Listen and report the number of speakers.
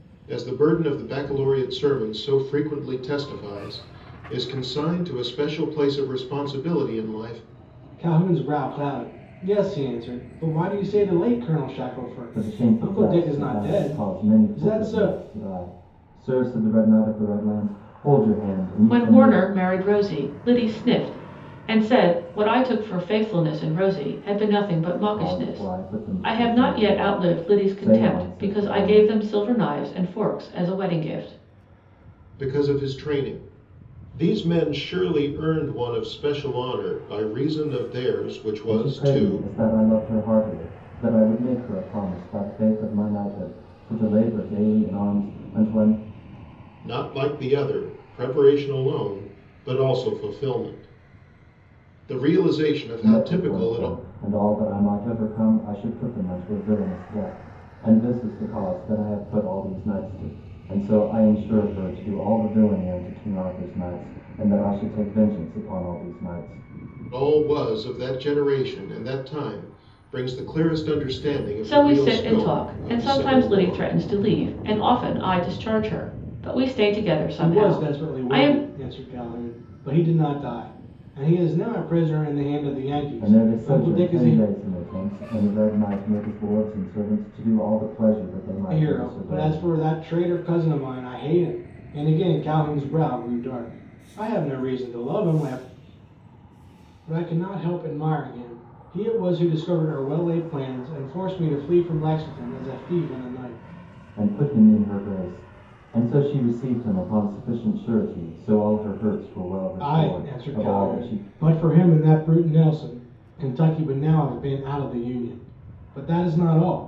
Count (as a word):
four